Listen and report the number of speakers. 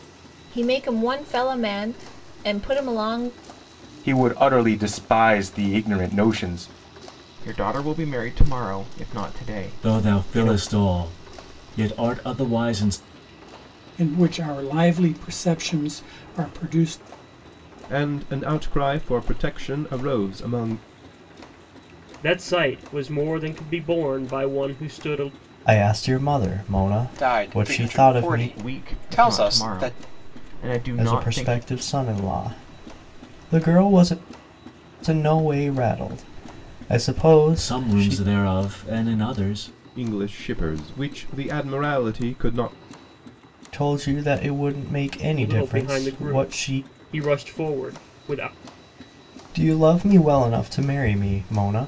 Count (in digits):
9